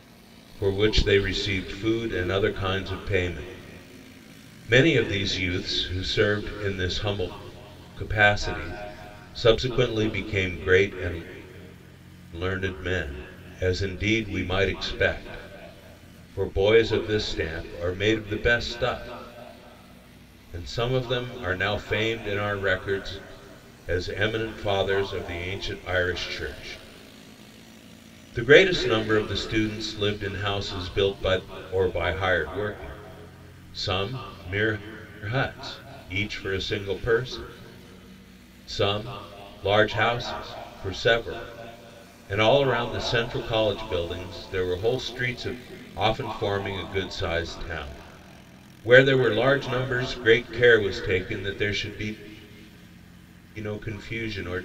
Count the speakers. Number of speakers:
one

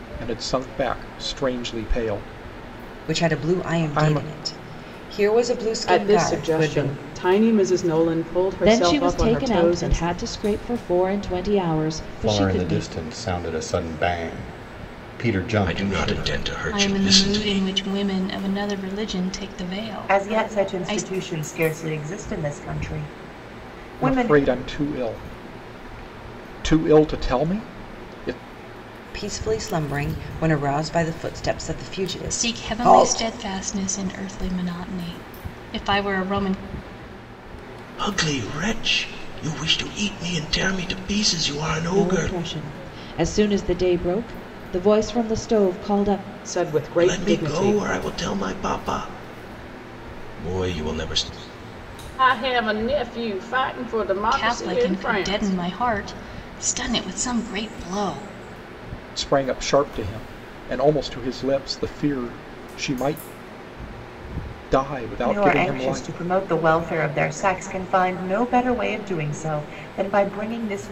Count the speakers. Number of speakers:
eight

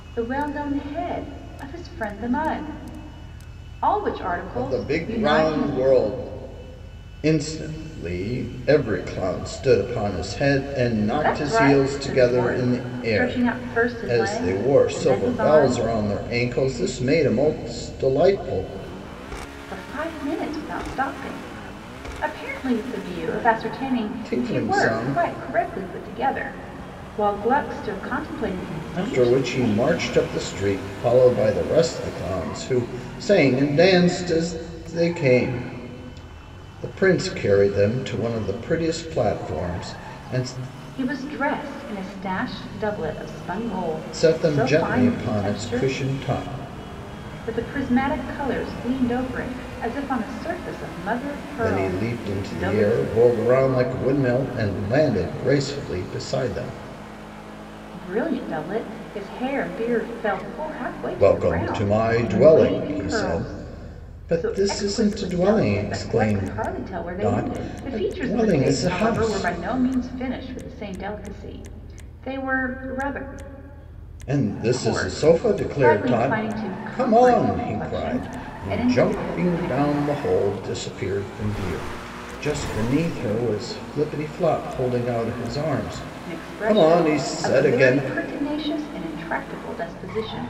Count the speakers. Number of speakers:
two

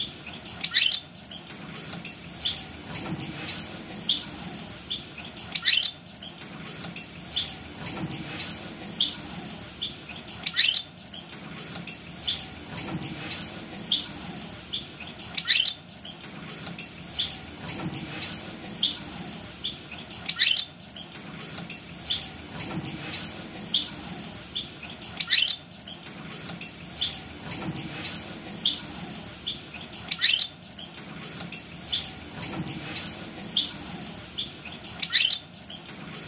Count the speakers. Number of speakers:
zero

